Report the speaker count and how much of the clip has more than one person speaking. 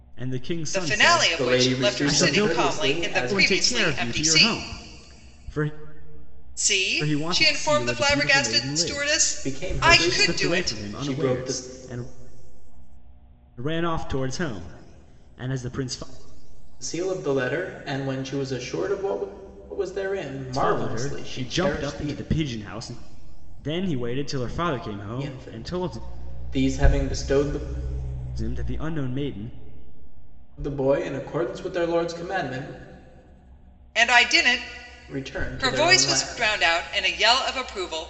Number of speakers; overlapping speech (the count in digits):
3, about 33%